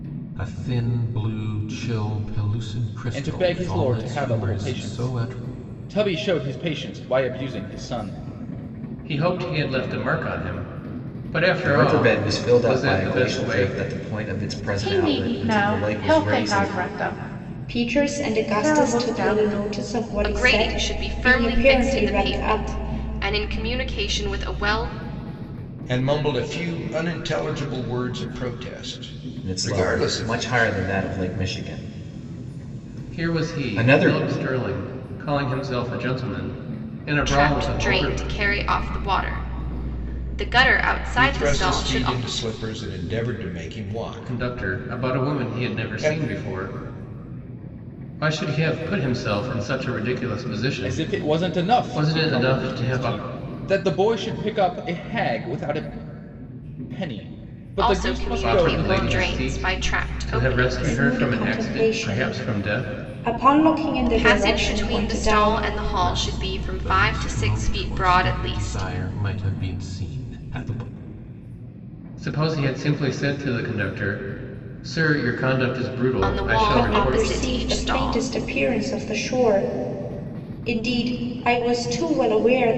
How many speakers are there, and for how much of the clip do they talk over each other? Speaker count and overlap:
8, about 38%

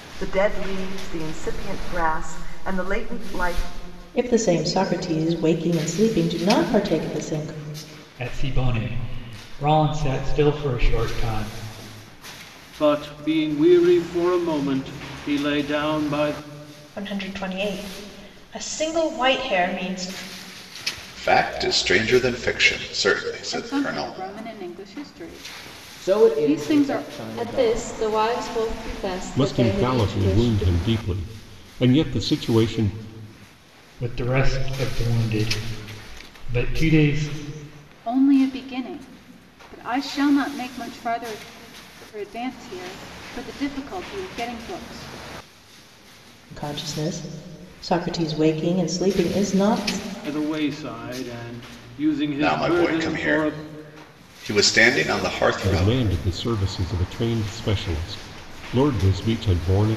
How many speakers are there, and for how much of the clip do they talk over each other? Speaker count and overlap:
10, about 9%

